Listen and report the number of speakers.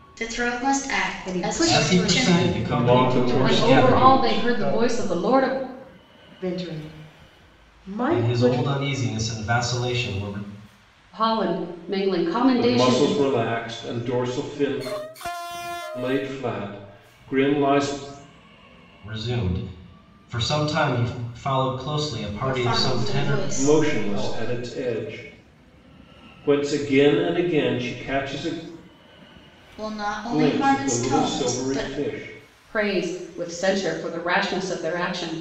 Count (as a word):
six